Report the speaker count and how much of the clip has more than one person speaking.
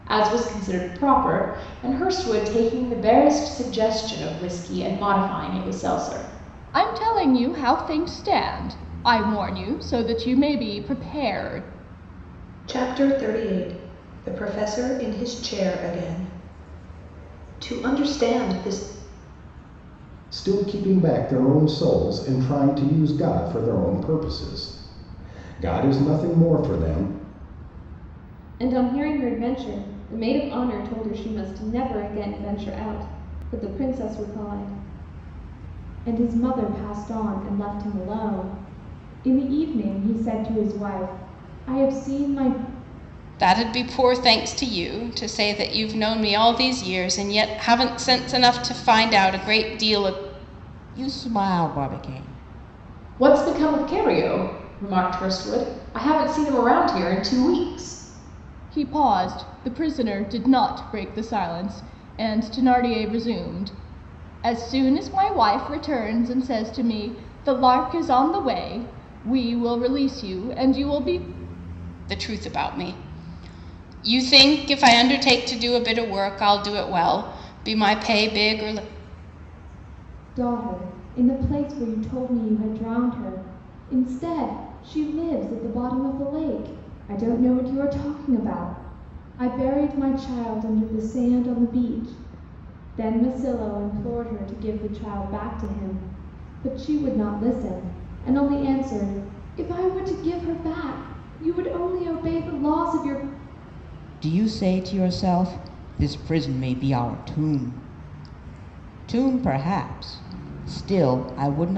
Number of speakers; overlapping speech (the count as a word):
eight, no overlap